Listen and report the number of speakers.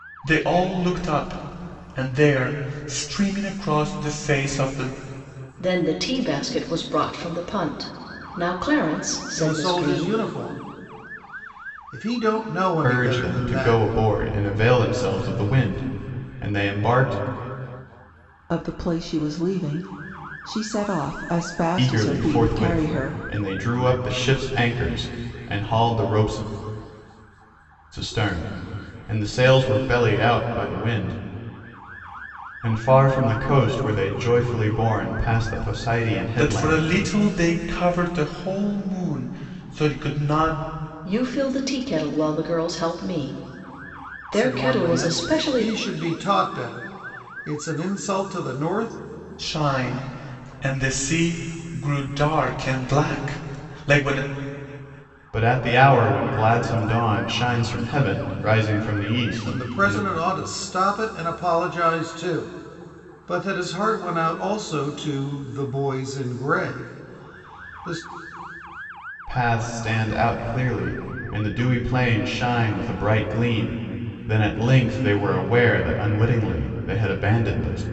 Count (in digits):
5